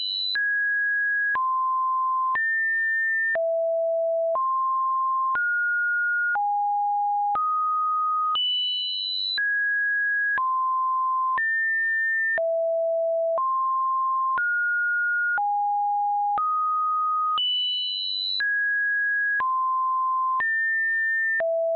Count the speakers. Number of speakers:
zero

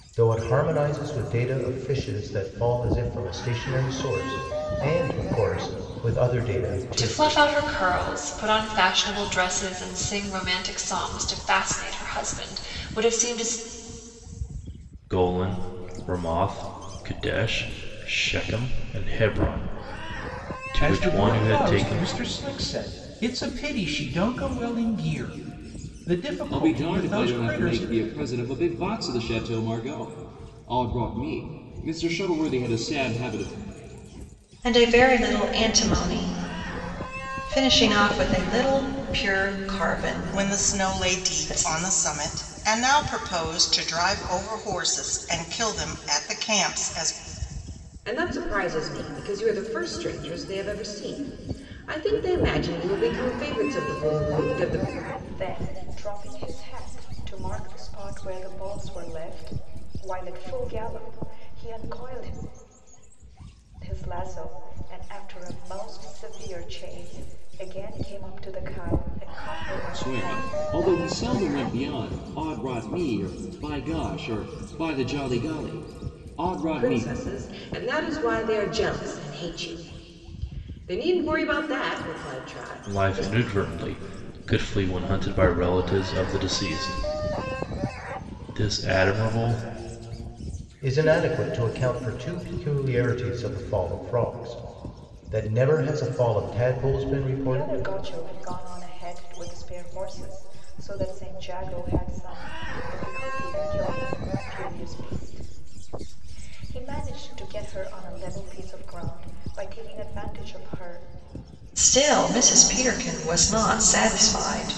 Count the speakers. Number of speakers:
nine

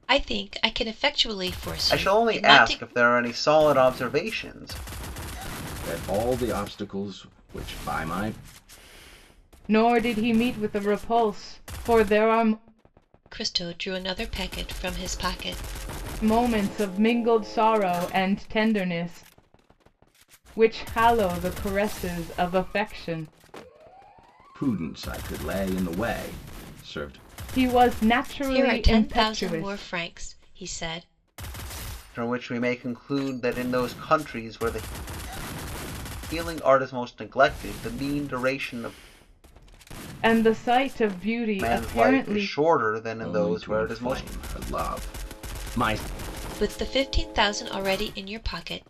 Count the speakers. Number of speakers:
four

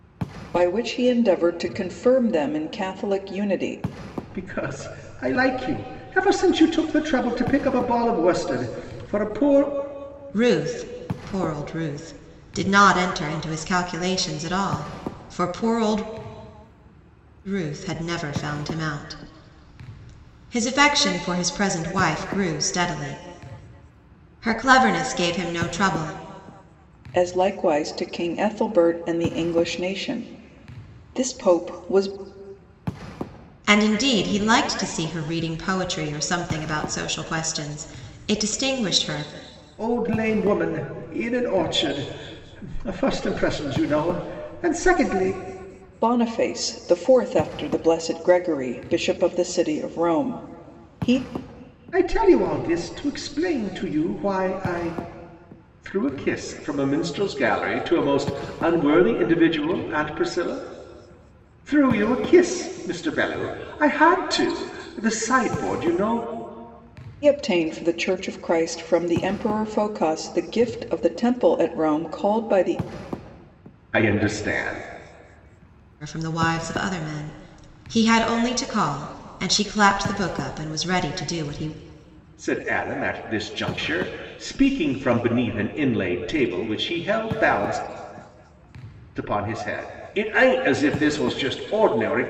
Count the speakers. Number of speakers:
three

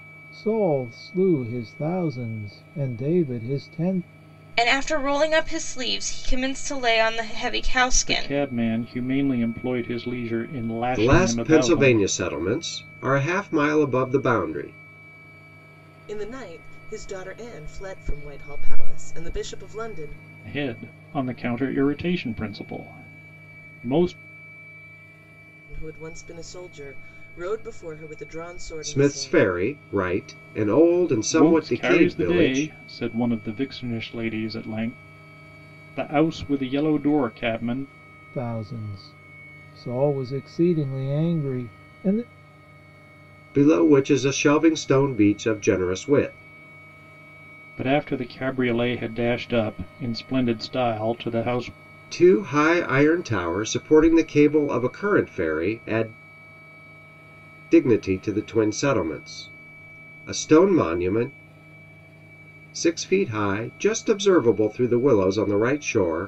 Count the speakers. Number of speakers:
five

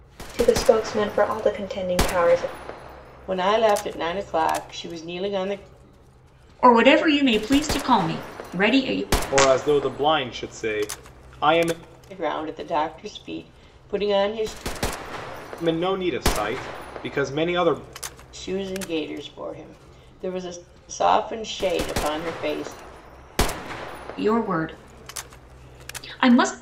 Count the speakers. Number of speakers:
four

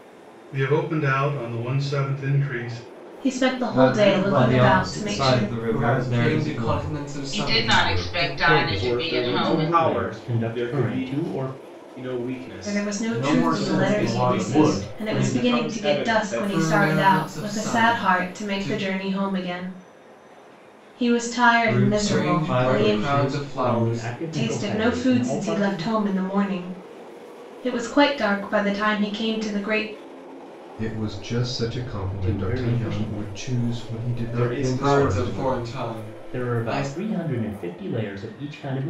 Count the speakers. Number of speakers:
nine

